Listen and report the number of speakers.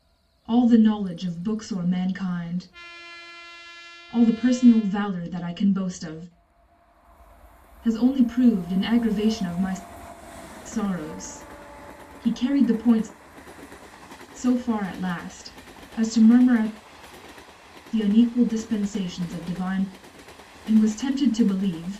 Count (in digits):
1